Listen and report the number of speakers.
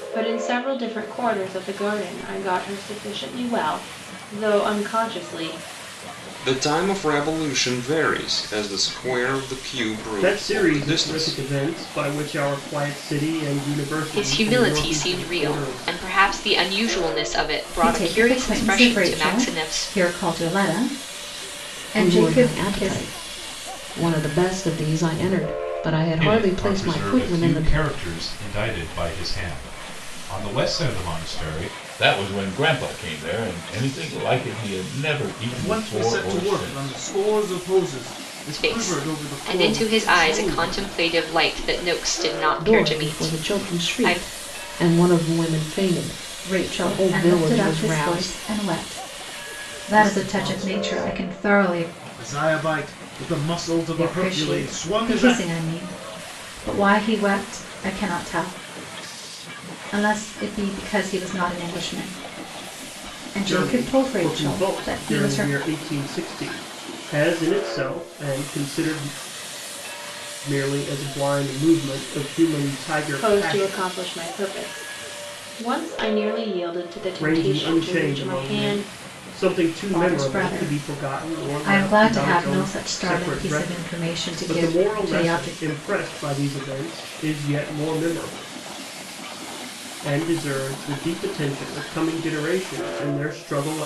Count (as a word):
nine